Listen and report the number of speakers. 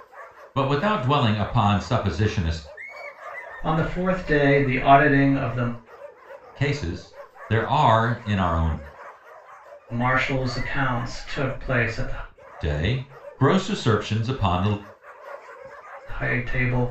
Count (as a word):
two